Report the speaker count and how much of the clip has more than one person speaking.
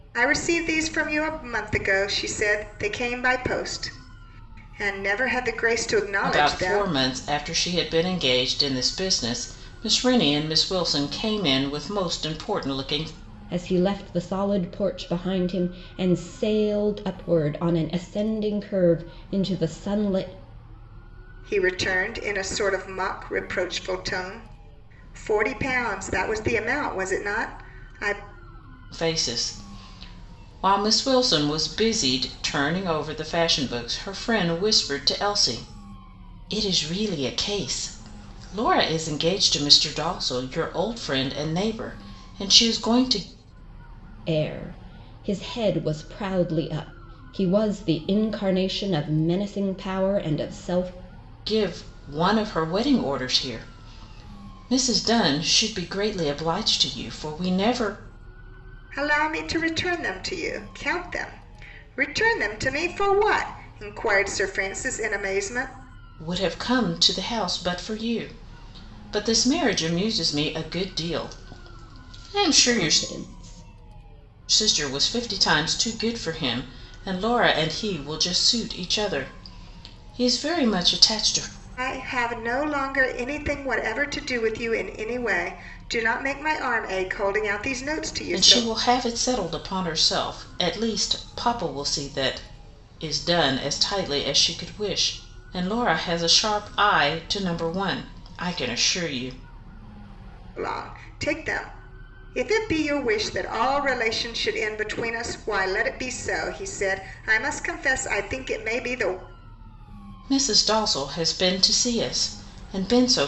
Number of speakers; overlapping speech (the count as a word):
three, about 1%